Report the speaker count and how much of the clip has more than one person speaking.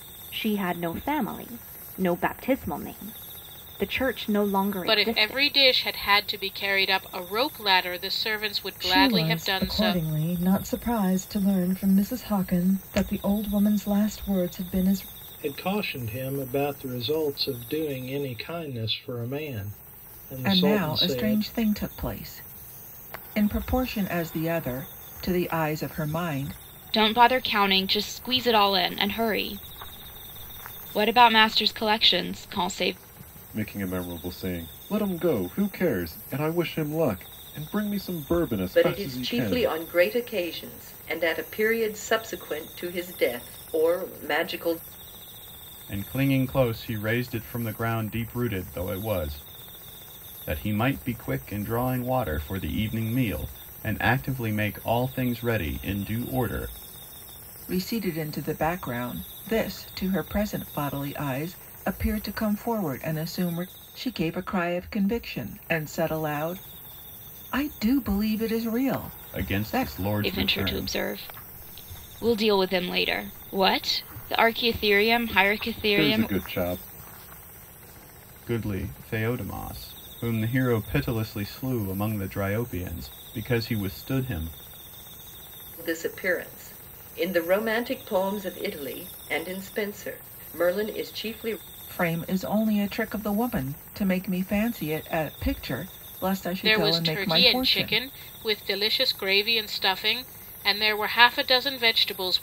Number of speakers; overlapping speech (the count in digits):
9, about 7%